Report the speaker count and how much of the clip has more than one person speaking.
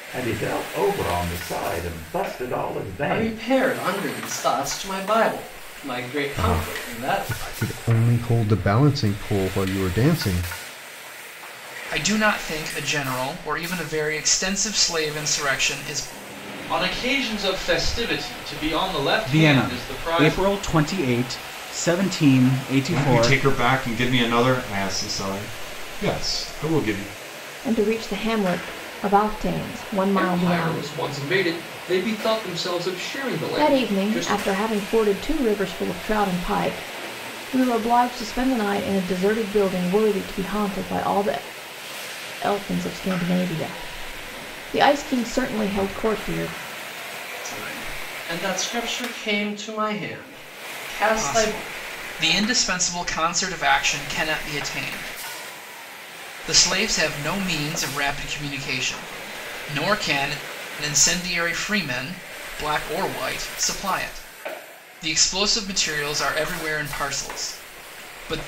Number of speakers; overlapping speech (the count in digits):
9, about 8%